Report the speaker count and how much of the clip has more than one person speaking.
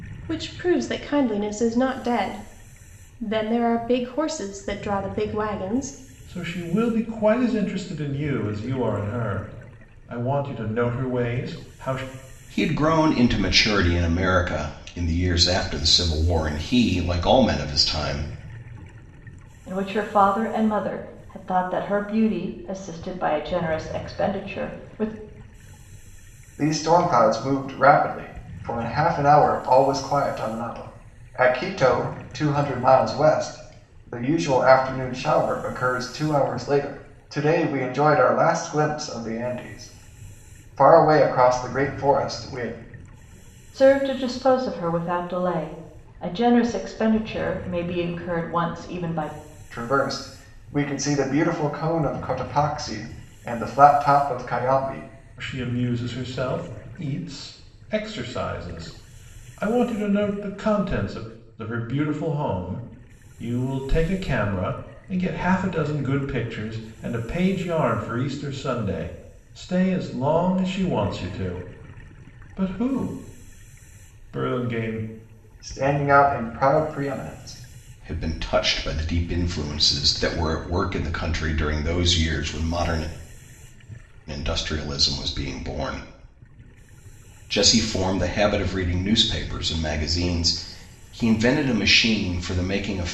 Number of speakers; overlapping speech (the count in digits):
5, no overlap